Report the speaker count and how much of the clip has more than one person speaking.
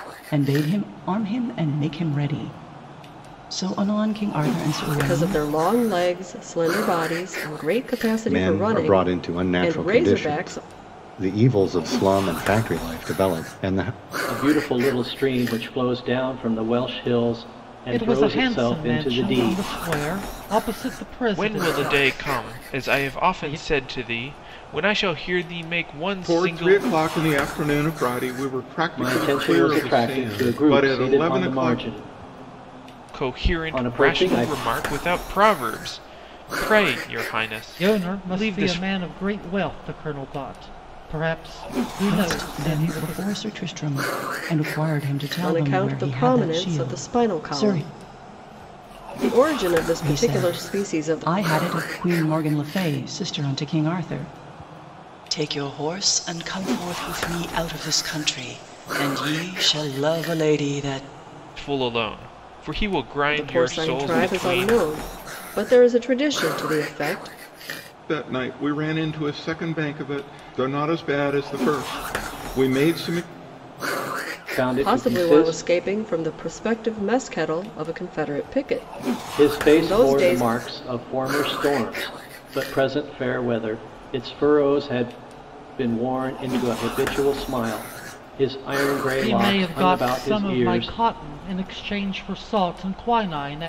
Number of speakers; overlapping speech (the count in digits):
7, about 25%